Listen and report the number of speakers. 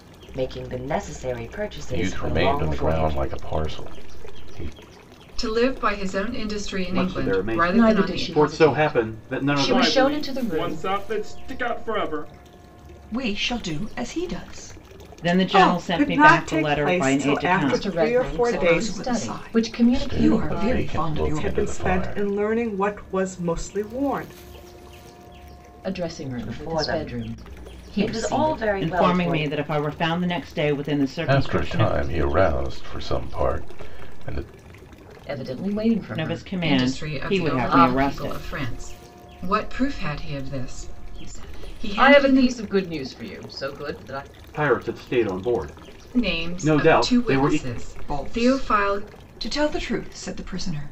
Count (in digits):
9